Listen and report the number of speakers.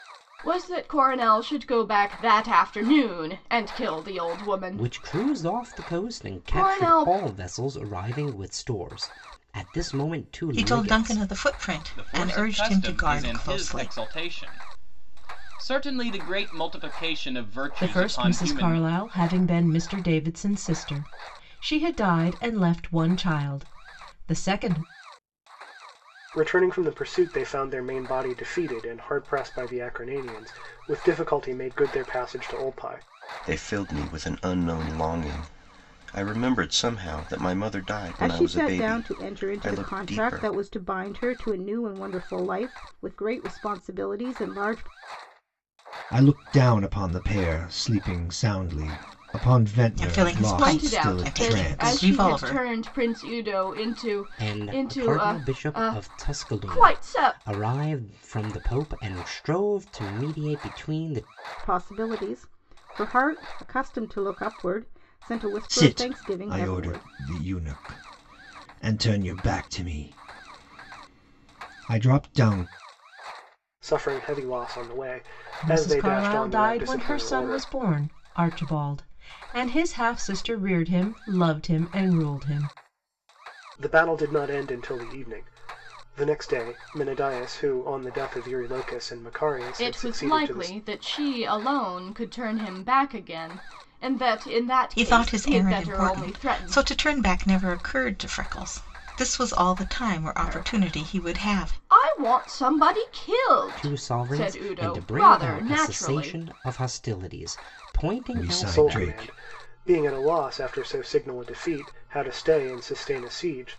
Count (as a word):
nine